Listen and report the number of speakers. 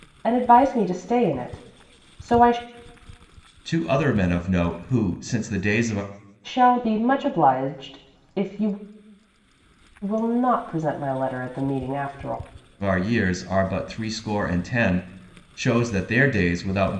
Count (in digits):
2